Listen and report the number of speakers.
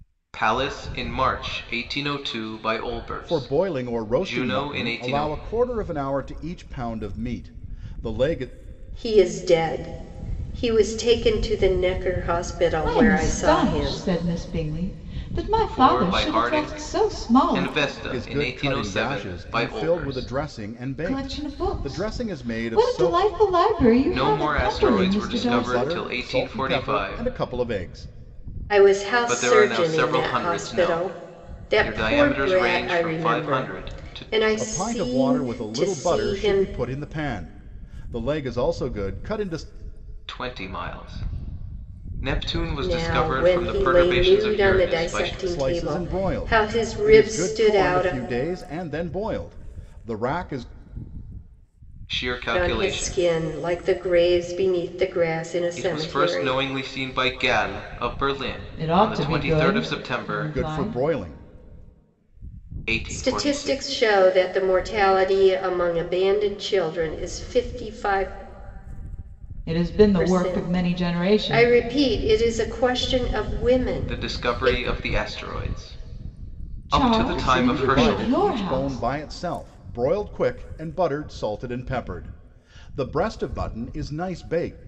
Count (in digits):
4